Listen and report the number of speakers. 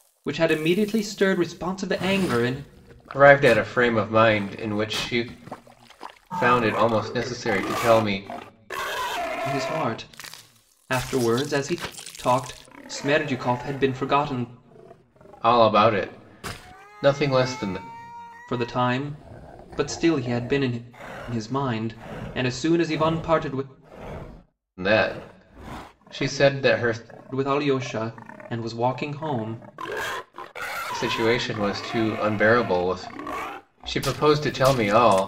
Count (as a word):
two